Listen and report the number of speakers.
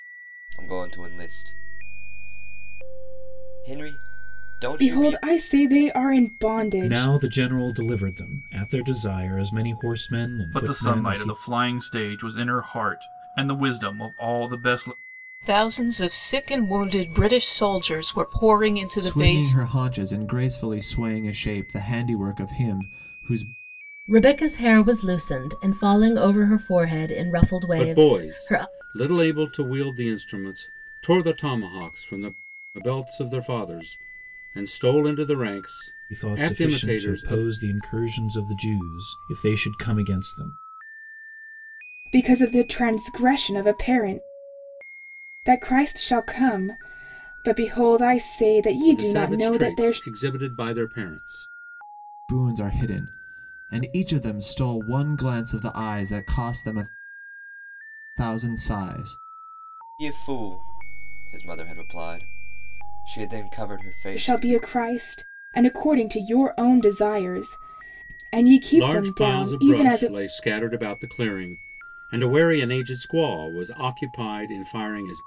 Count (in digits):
8